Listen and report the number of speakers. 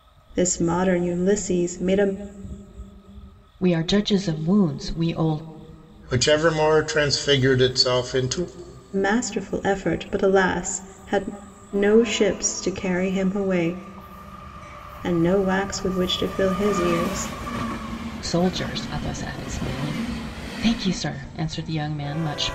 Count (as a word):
three